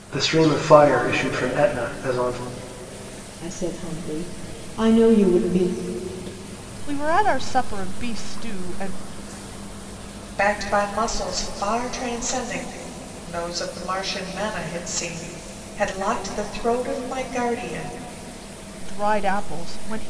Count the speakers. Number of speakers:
4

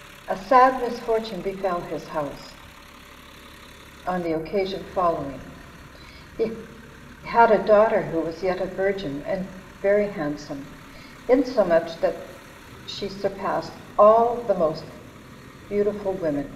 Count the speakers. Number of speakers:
1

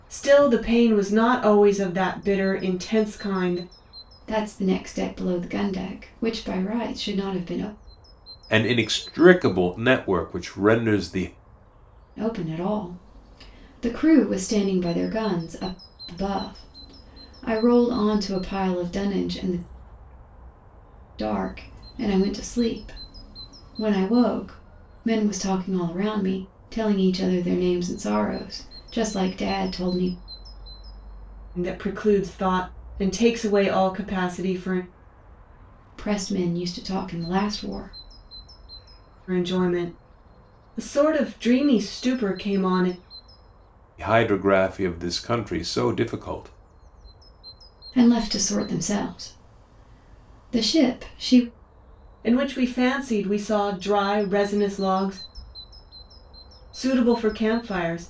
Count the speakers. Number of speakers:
3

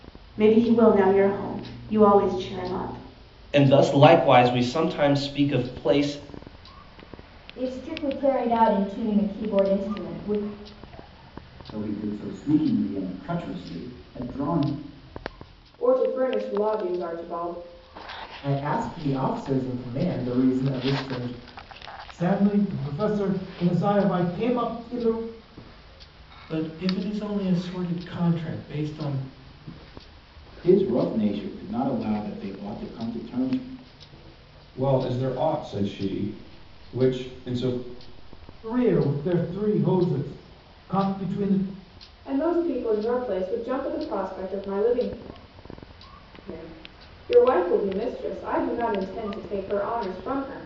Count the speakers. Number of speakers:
10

